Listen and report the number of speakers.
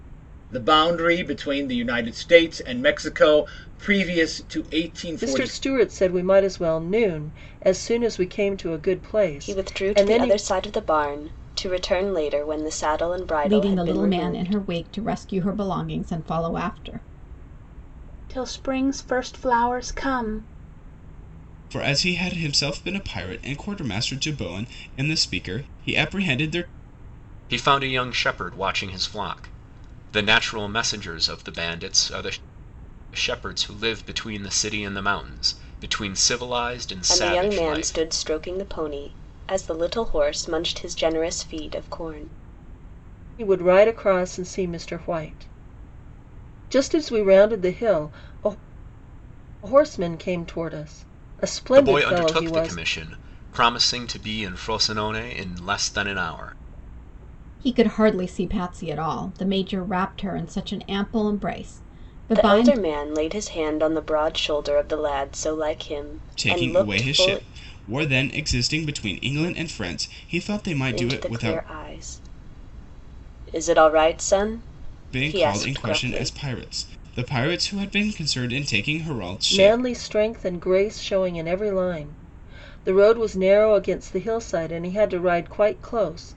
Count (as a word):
seven